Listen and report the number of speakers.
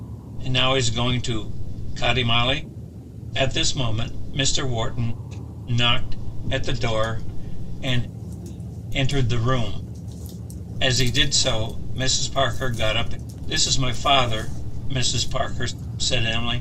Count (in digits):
1